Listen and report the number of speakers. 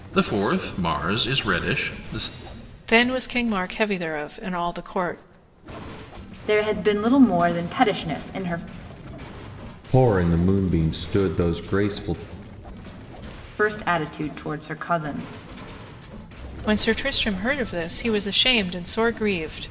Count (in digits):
4